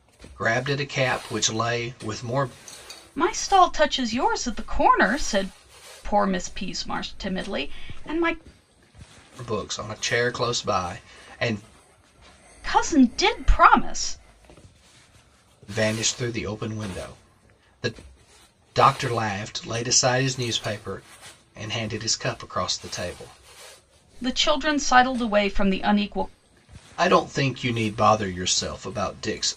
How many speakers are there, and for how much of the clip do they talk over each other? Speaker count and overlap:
2, no overlap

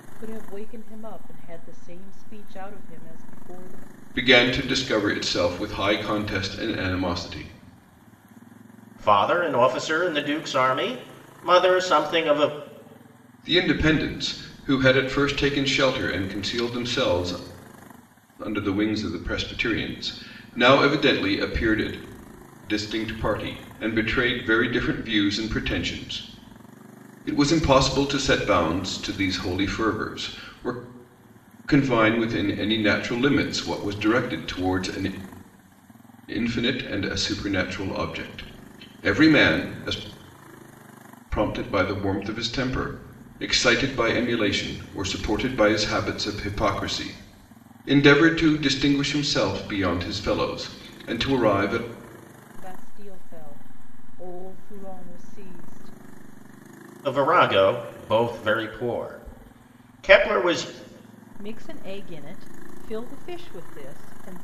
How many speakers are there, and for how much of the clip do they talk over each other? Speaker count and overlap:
3, no overlap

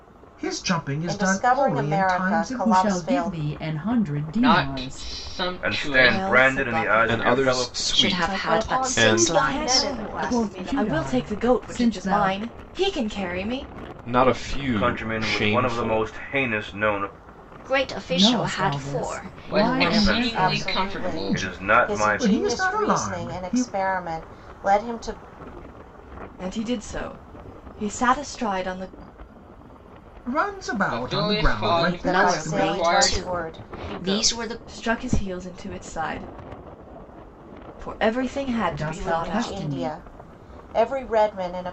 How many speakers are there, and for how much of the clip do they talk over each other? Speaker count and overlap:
9, about 52%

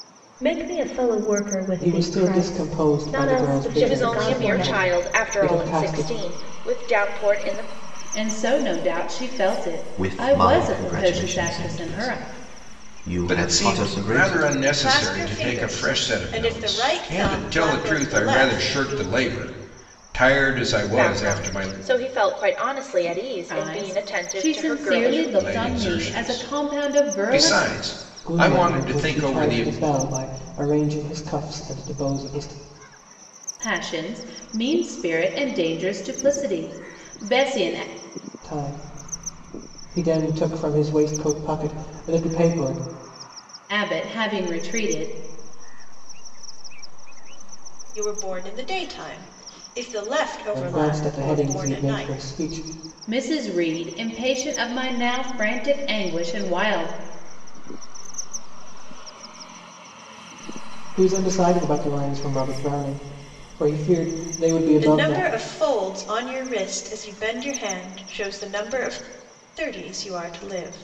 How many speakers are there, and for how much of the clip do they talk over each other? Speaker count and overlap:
8, about 42%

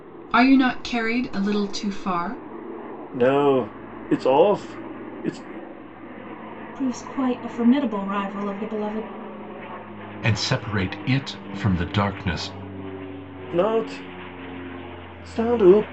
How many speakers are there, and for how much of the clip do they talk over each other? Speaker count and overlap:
4, no overlap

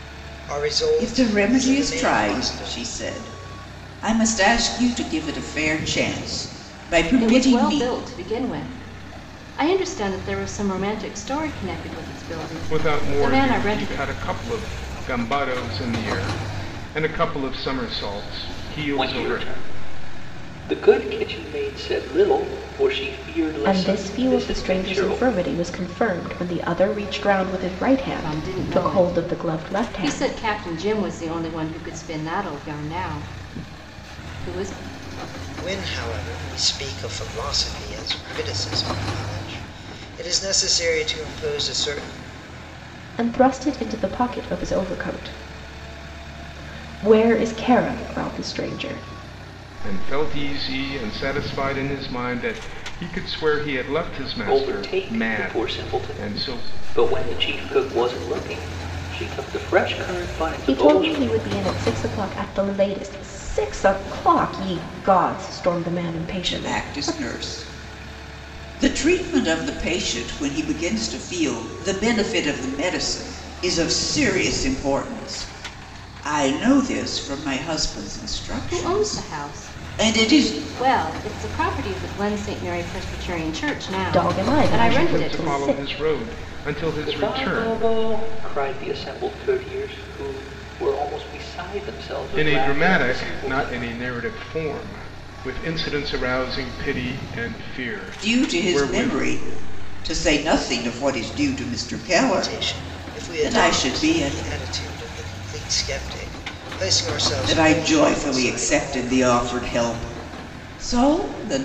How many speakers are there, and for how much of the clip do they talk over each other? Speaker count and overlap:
6, about 22%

